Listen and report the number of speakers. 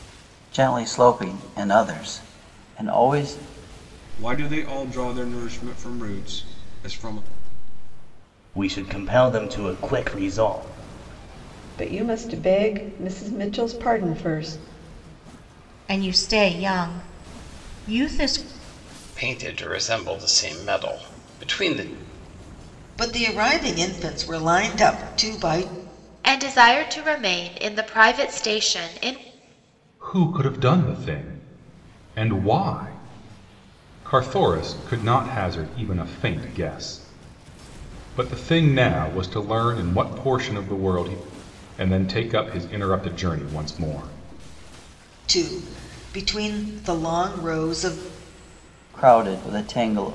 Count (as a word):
nine